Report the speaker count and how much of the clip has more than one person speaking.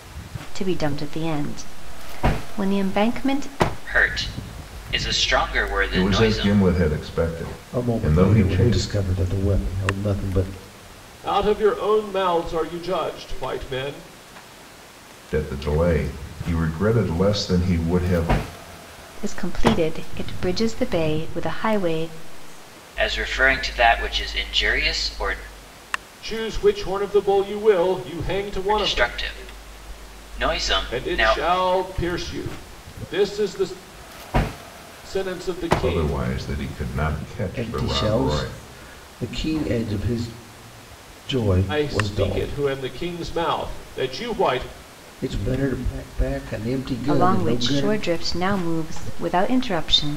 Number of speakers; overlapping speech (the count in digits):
5, about 13%